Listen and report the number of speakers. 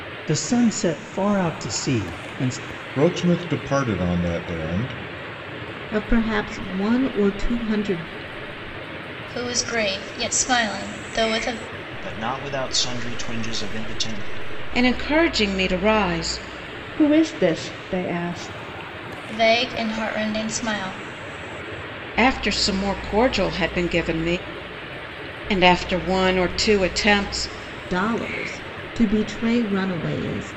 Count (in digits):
7